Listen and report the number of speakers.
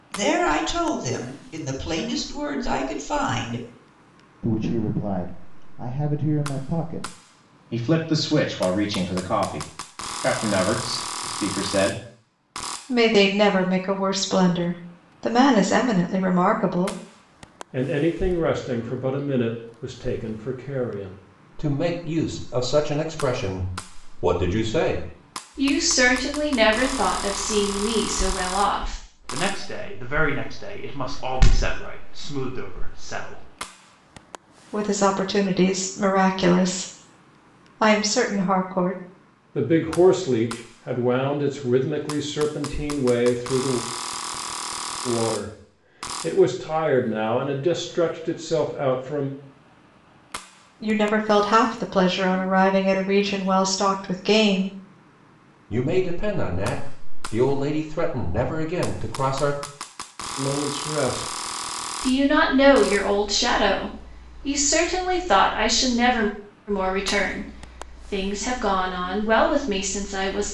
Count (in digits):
8